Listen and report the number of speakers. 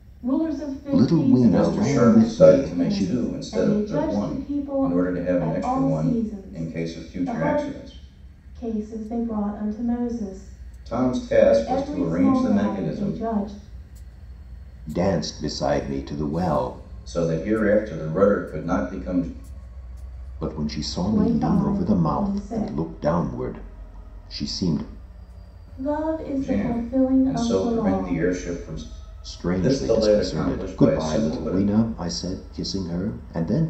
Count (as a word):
three